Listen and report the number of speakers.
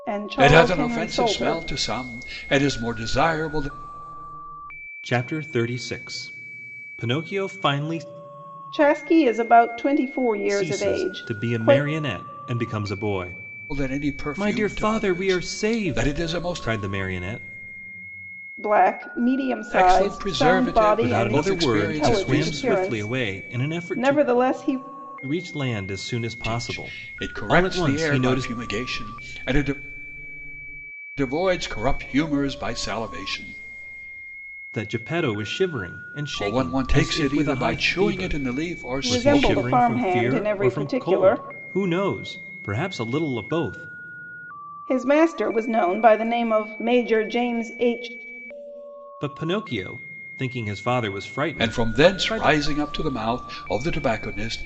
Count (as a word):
three